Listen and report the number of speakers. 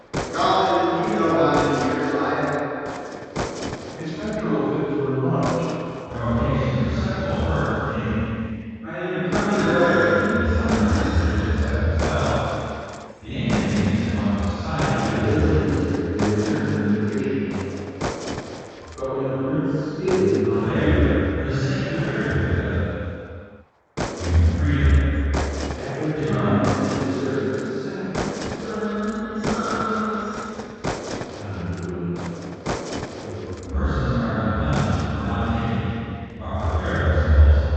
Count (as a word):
five